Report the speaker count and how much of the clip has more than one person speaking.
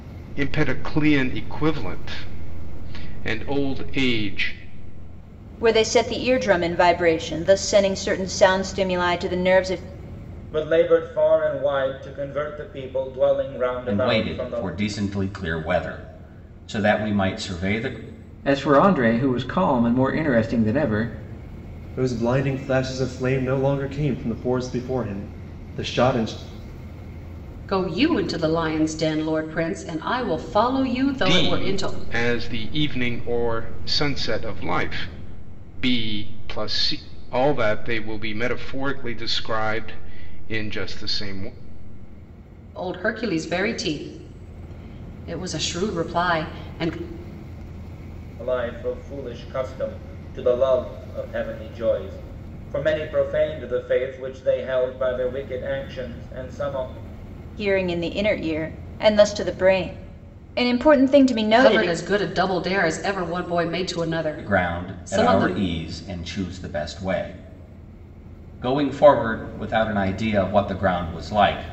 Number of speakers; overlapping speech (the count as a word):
seven, about 4%